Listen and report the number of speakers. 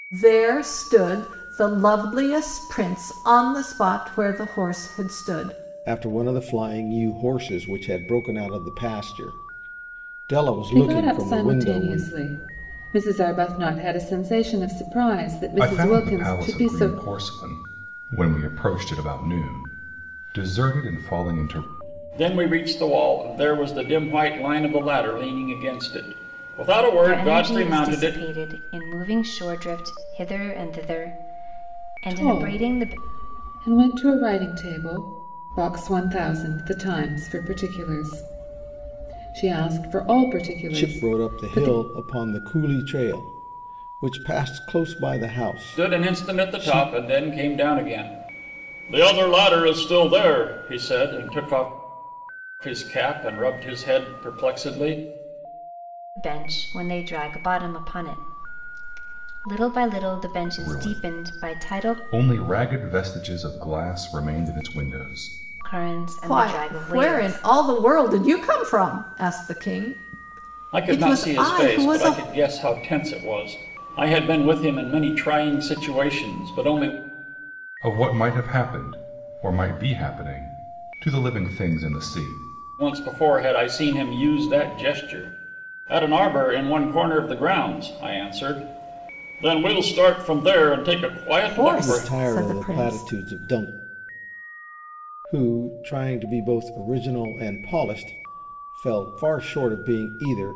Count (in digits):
6